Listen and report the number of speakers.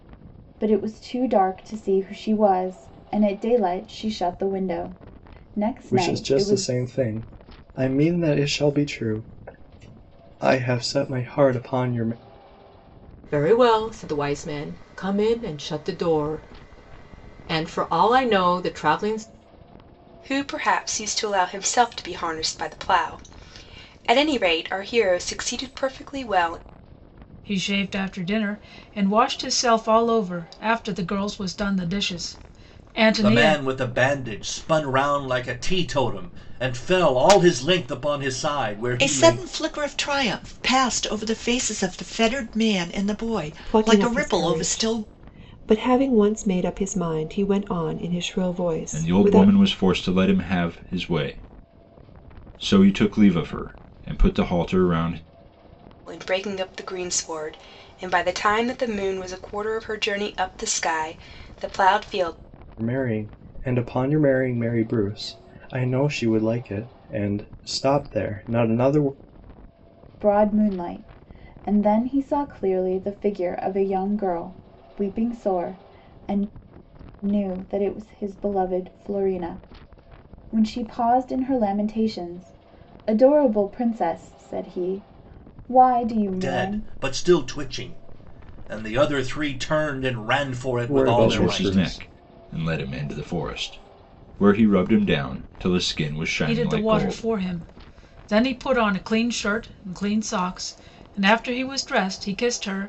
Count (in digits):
9